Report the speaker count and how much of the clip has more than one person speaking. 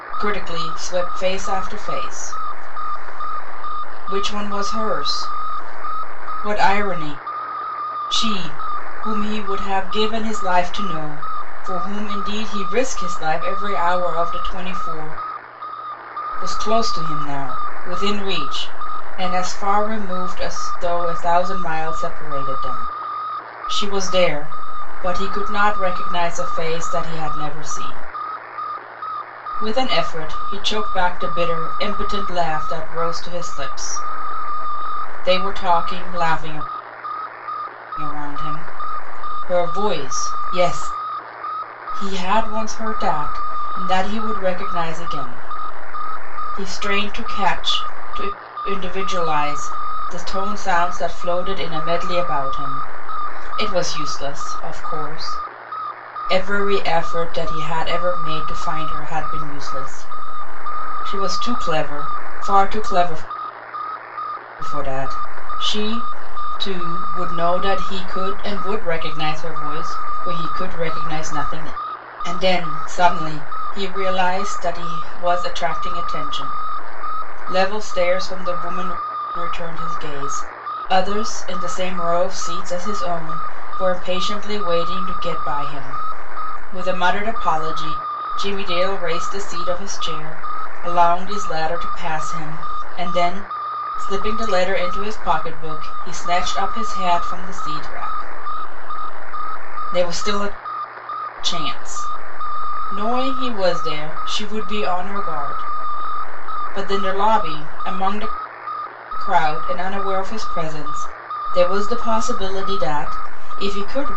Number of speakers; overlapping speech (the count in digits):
1, no overlap